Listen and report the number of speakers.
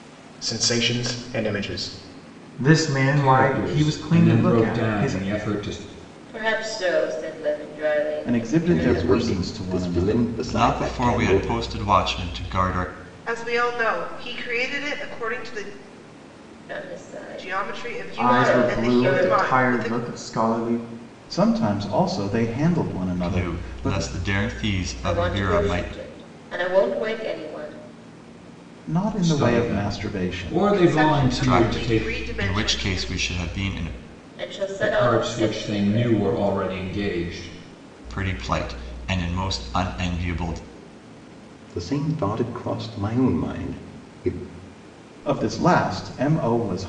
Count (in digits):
8